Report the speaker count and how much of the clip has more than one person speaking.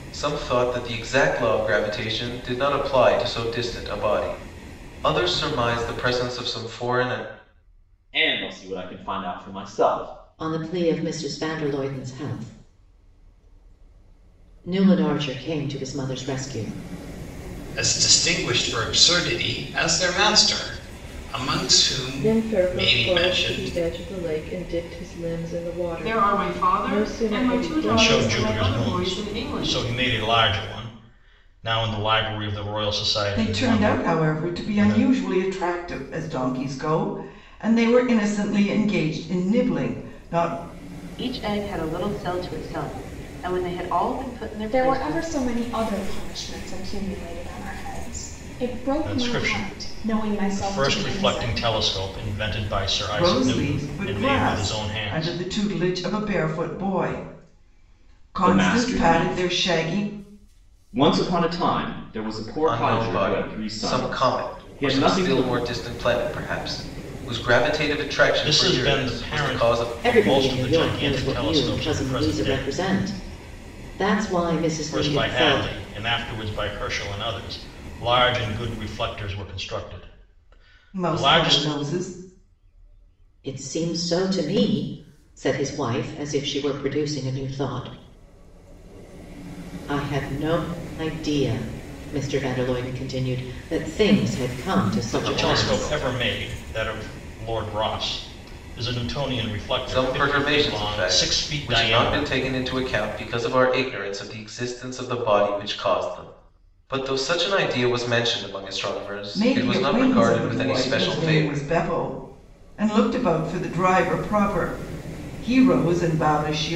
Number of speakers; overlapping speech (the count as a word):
ten, about 25%